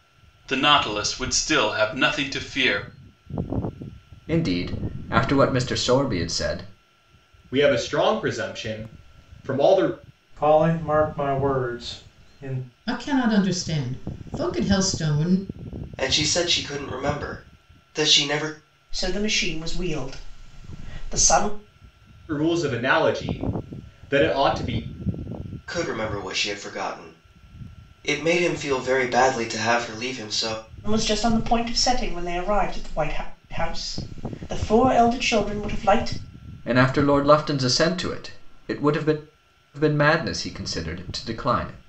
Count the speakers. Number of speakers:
7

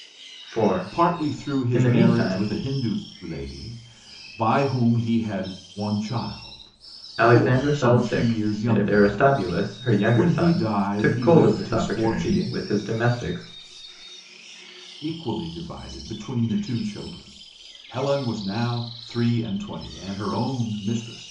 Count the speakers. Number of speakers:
2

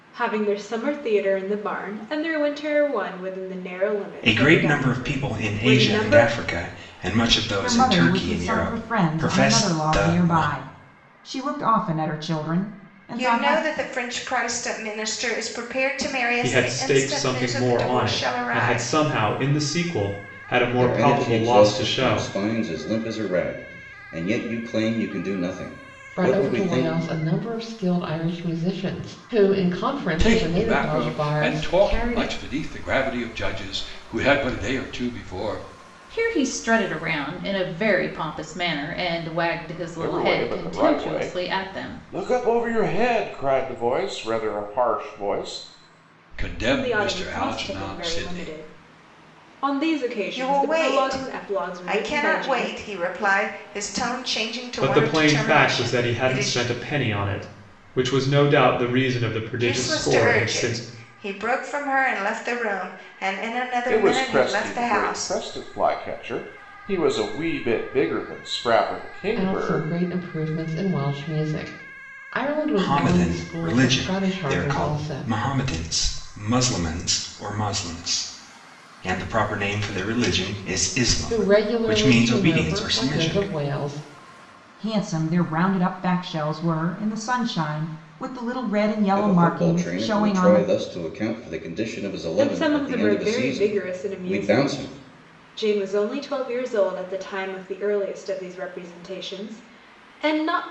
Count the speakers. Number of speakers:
10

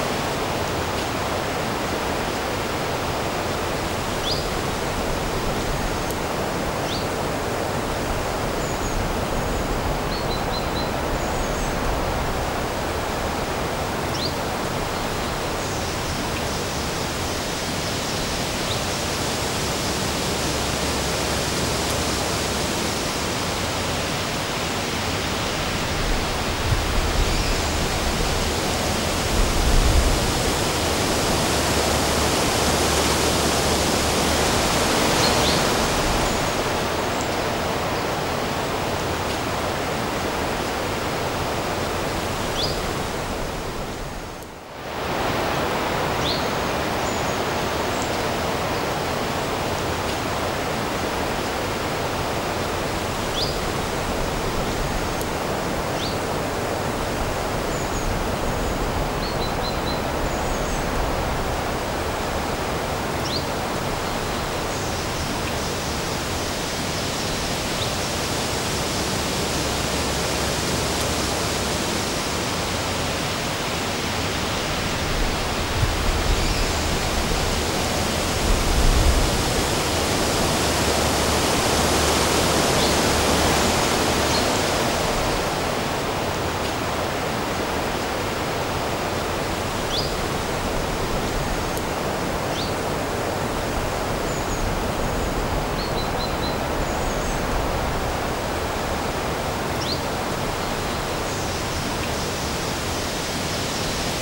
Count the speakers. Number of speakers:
0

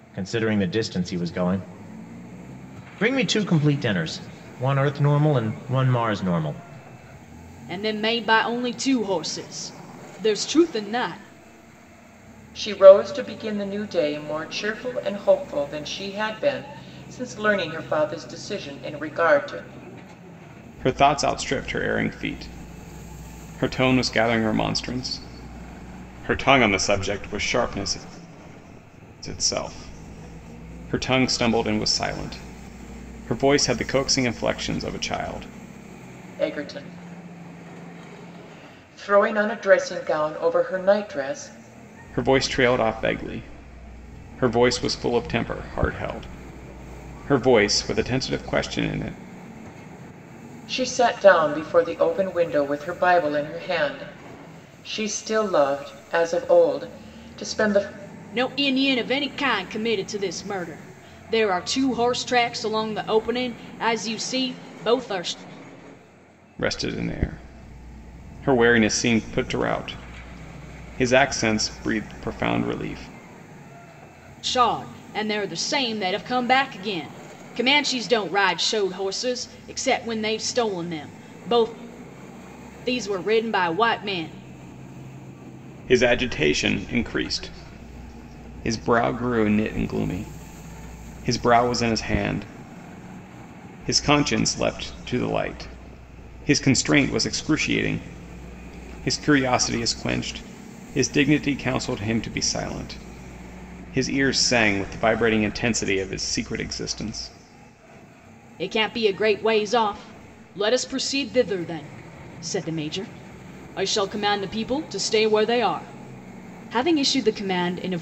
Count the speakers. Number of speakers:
4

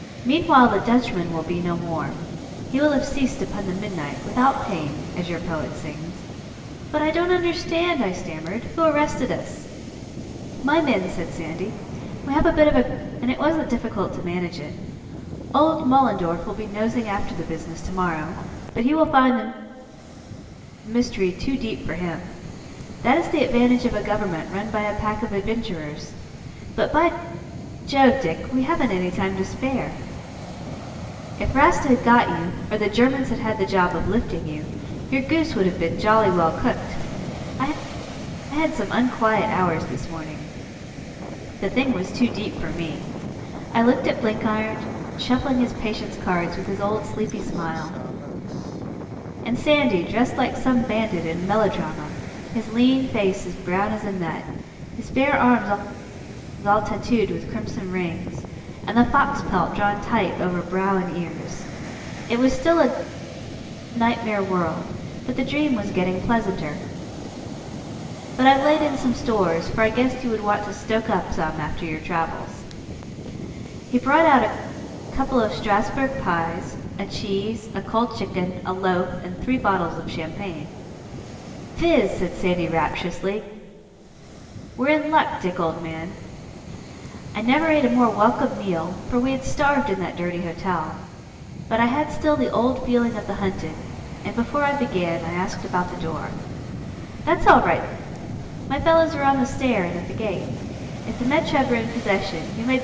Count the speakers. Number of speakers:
1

